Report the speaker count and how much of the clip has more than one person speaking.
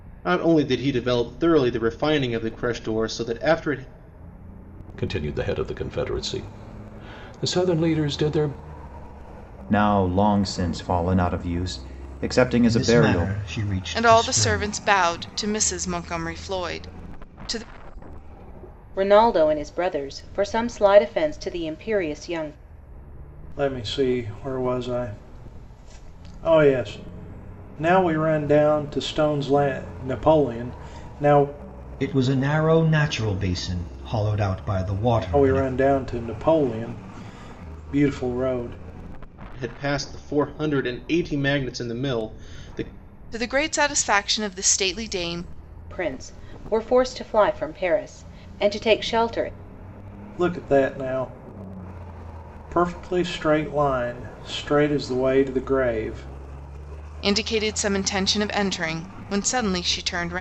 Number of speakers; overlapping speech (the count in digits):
7, about 3%